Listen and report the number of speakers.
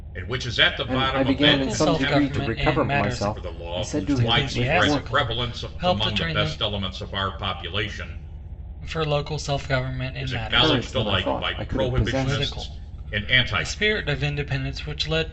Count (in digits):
3